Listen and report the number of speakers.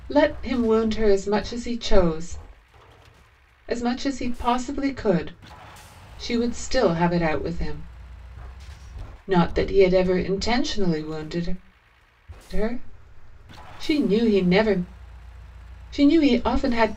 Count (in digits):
1